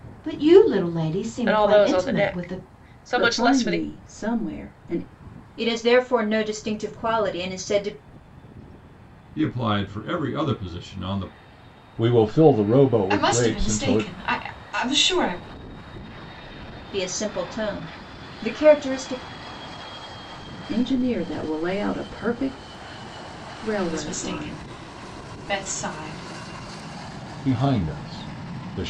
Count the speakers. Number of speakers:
7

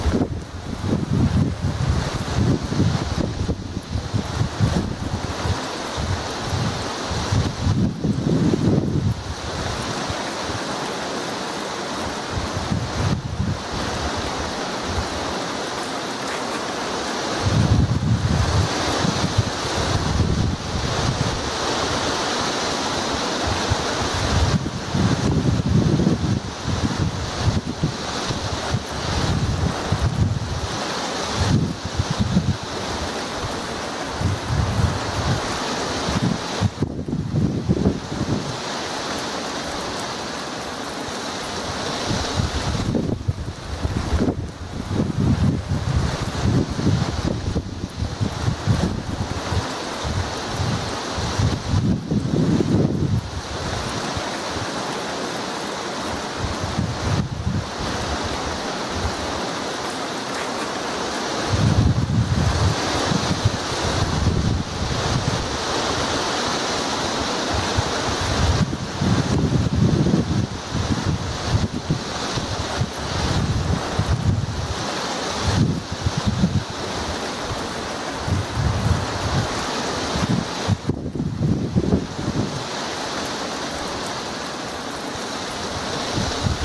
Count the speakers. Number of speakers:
0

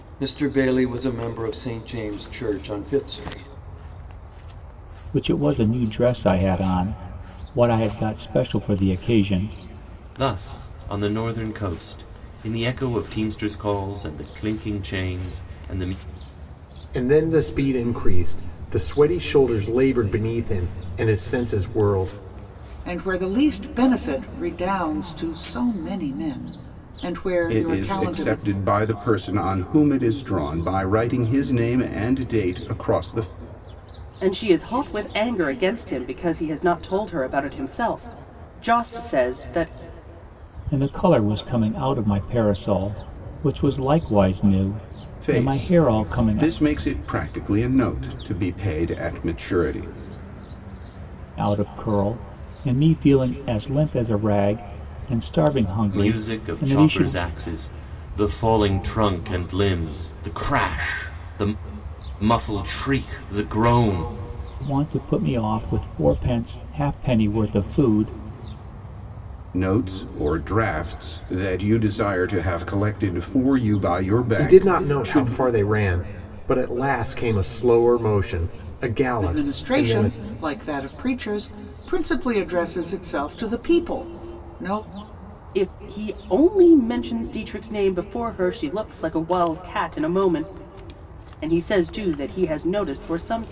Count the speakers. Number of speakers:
7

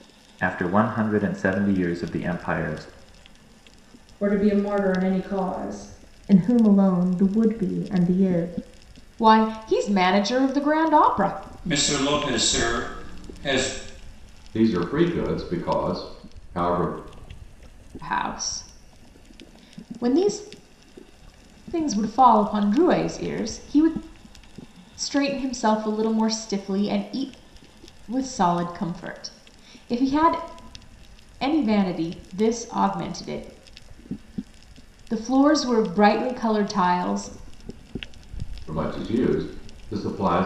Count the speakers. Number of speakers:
6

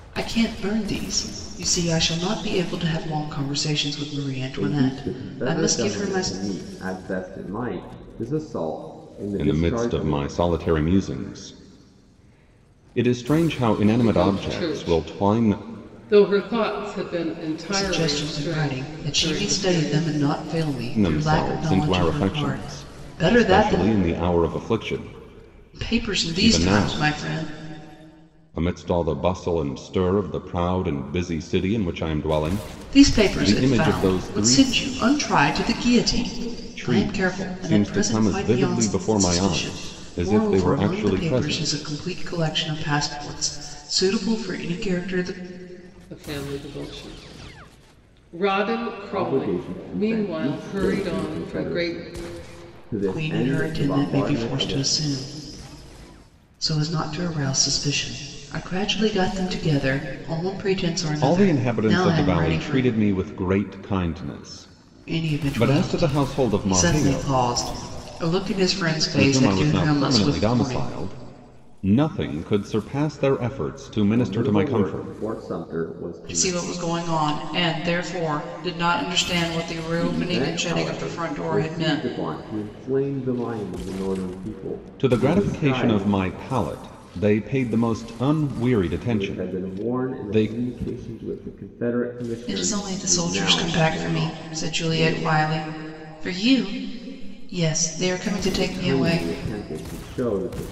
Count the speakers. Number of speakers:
4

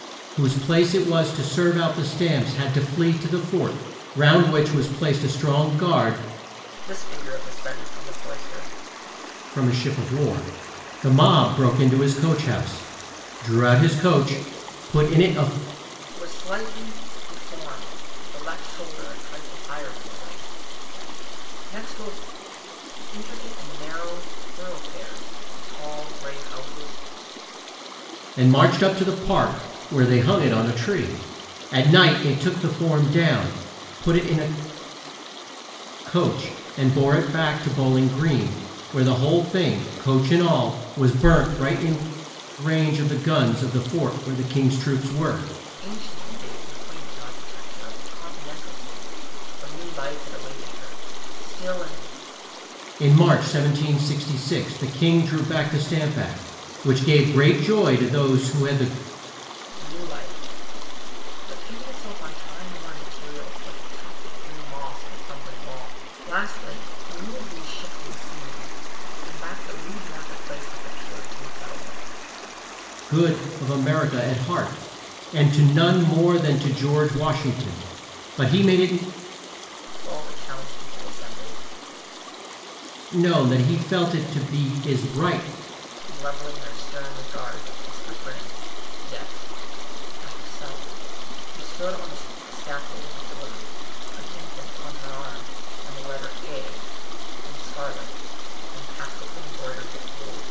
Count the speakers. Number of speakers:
2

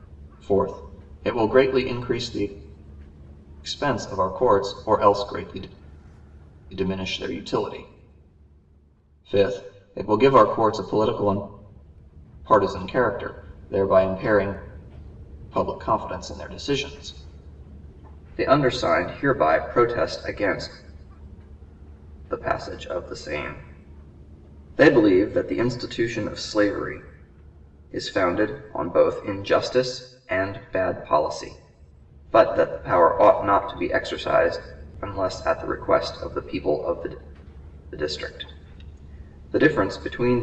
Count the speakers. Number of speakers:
1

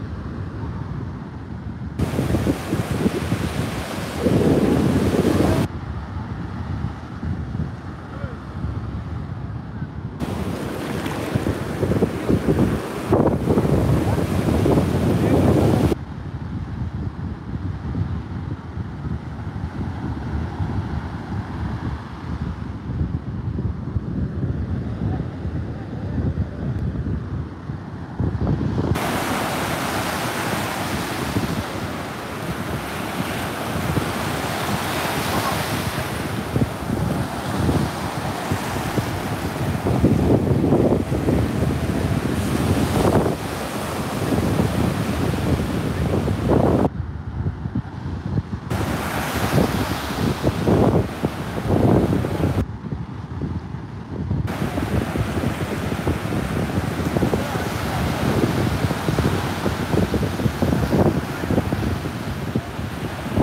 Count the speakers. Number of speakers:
0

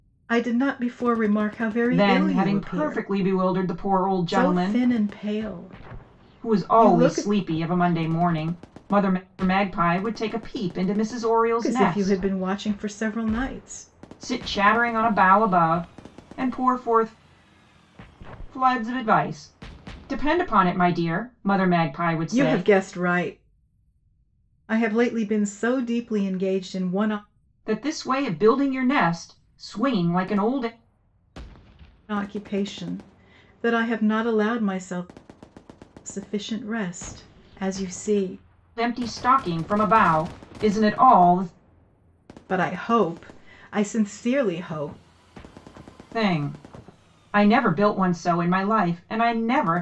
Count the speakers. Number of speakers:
2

